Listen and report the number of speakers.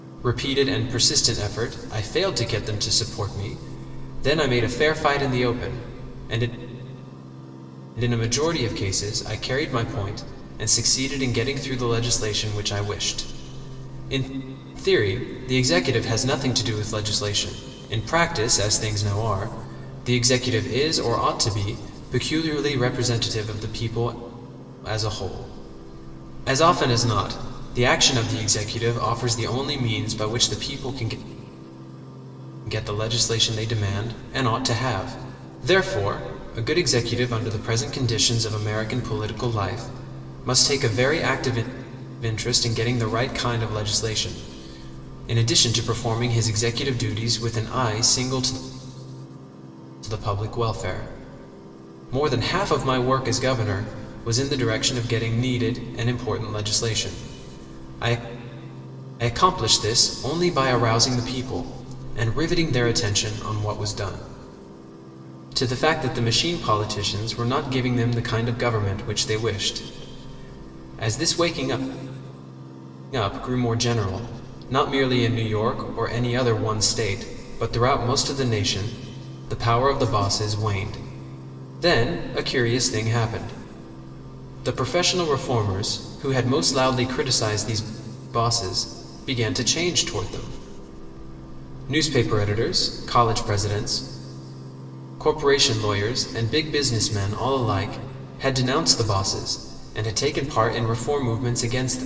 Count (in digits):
1